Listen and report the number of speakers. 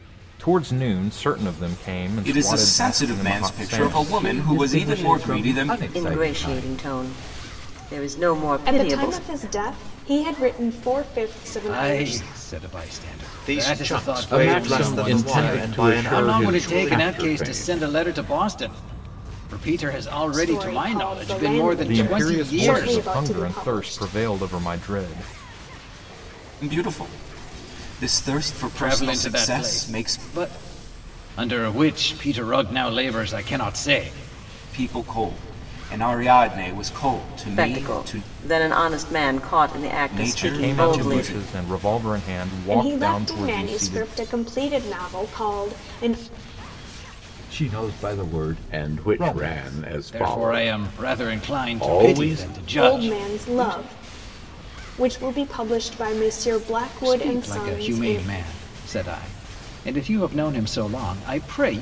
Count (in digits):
8